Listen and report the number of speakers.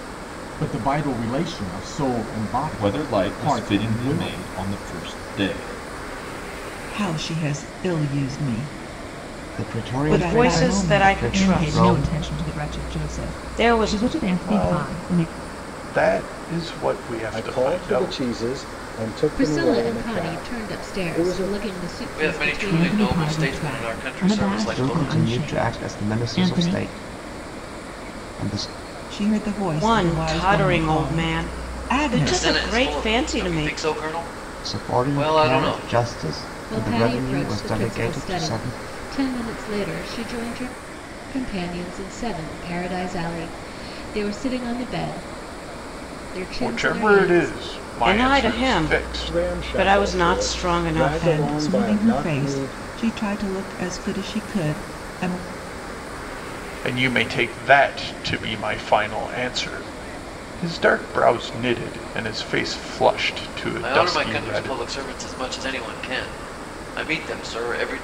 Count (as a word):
ten